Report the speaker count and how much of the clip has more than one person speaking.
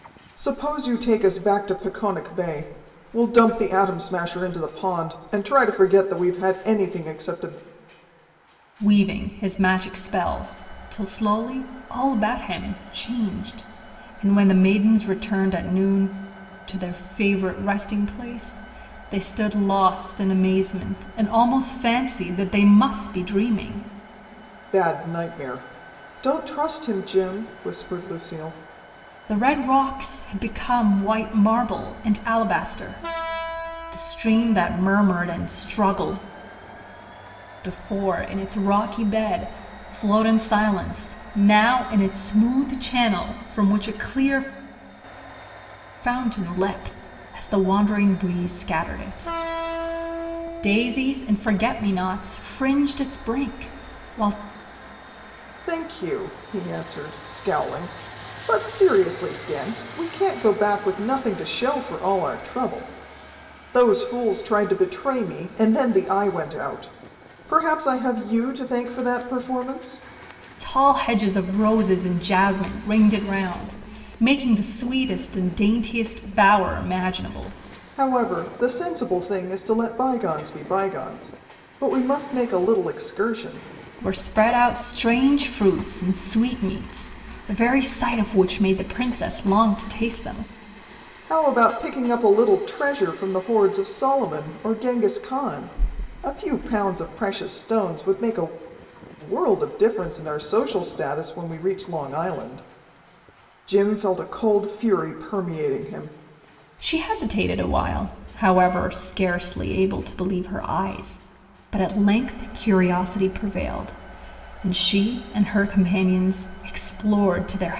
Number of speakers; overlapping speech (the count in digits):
2, no overlap